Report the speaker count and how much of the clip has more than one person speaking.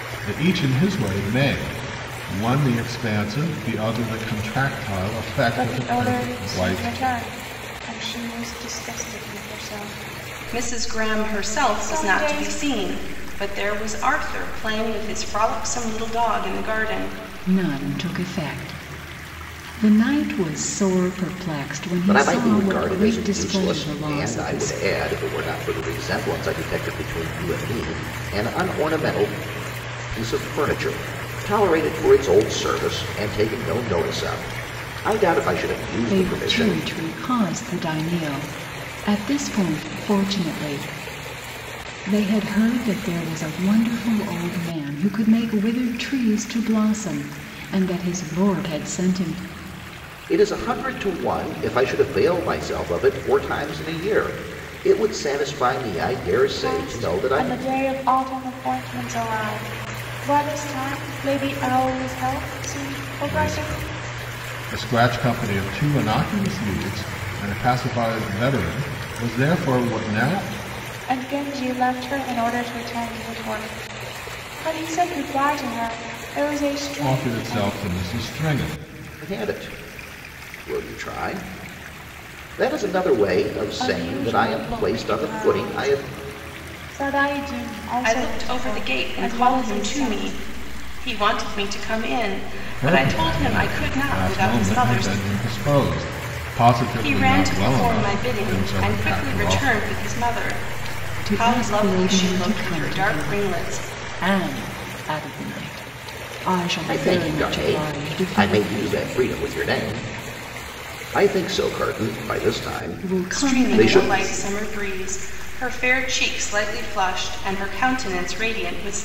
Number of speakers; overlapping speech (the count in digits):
5, about 21%